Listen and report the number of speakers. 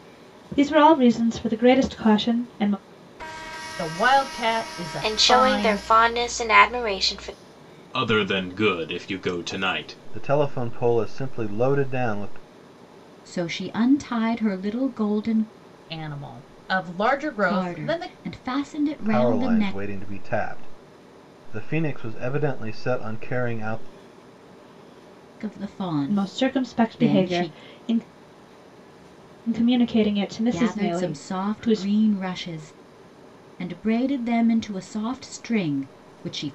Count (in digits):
6